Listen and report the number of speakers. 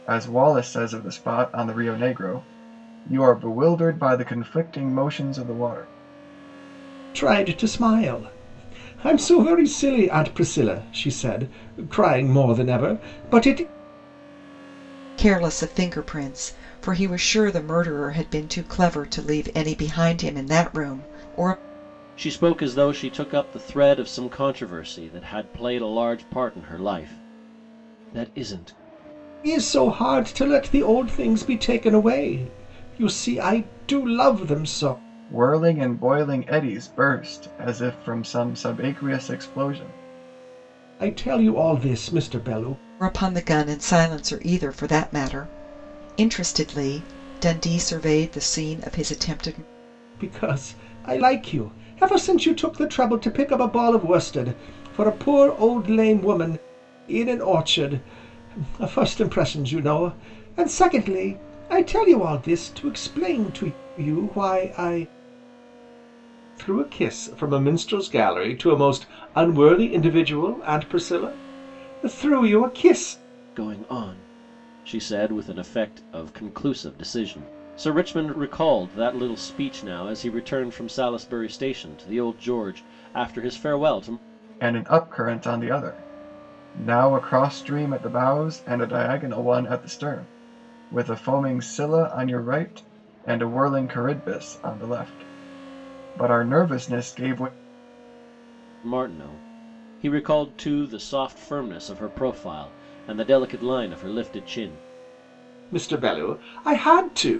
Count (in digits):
4